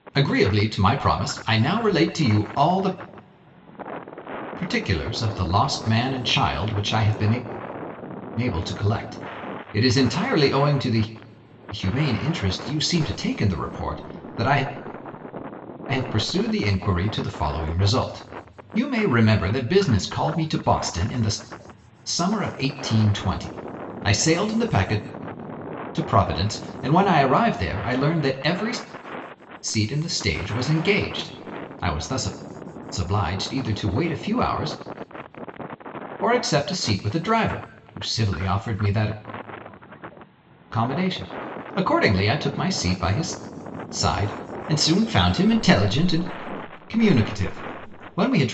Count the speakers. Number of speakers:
1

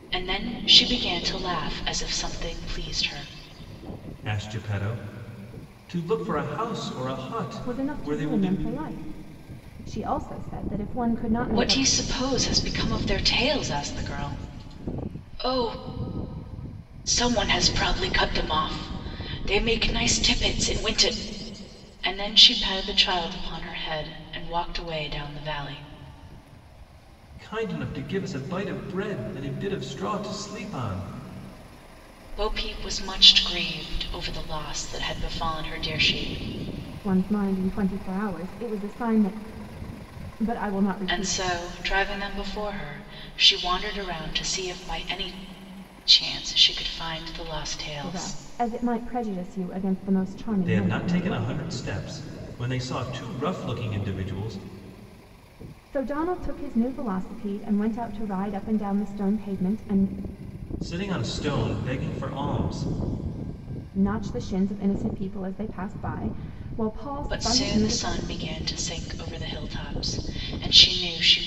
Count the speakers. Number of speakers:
3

